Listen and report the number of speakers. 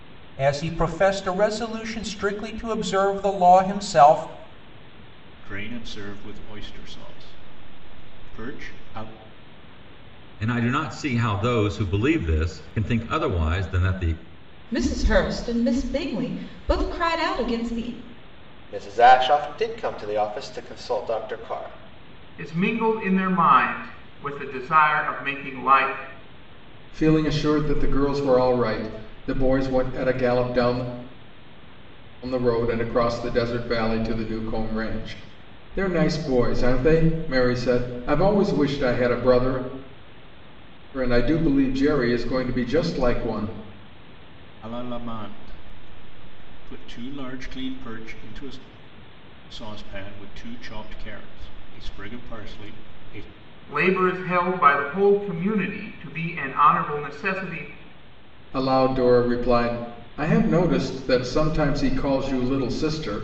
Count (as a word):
seven